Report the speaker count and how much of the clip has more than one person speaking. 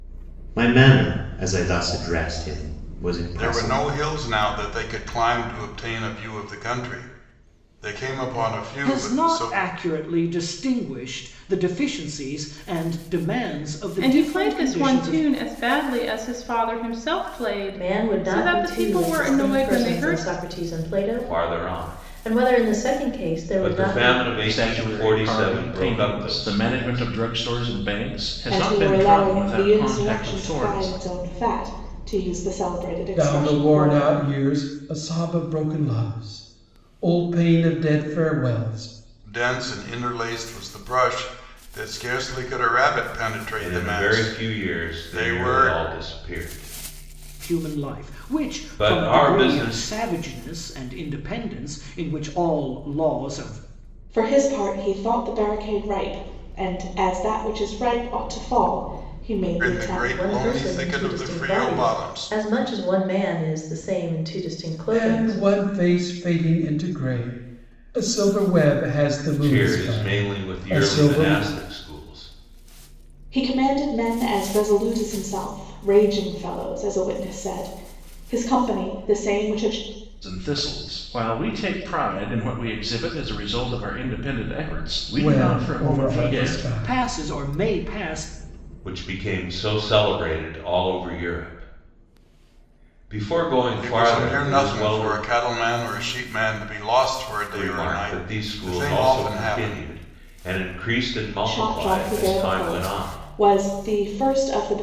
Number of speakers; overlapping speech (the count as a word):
nine, about 30%